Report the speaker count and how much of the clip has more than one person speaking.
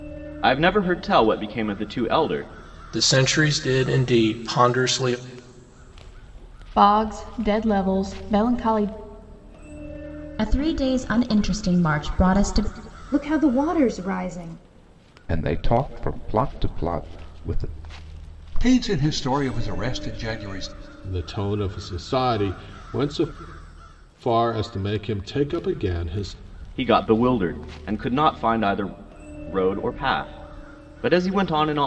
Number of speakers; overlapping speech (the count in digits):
8, no overlap